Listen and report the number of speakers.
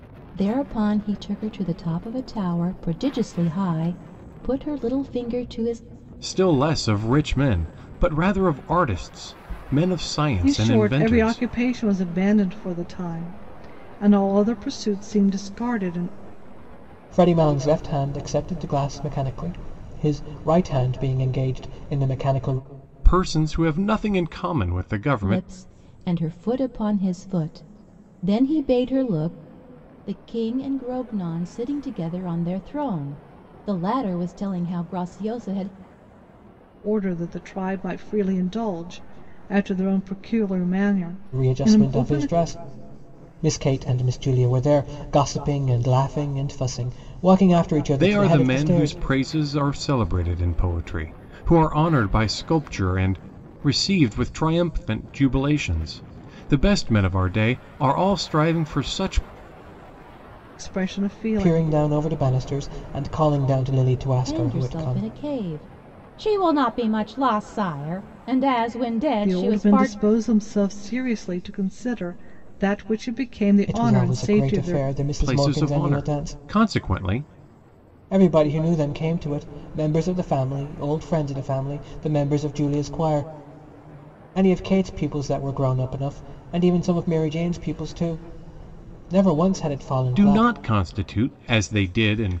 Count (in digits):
4